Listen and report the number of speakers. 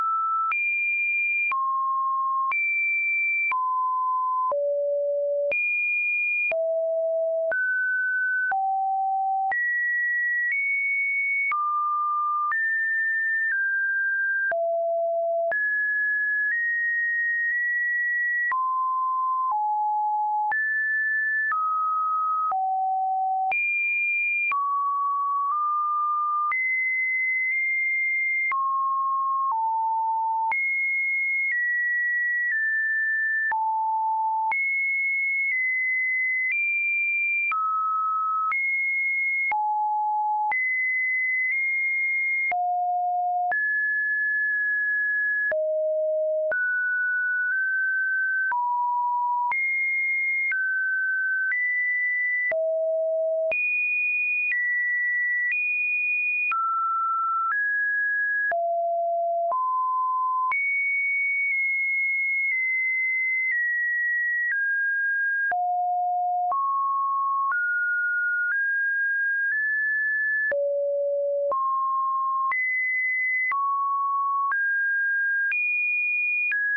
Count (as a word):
zero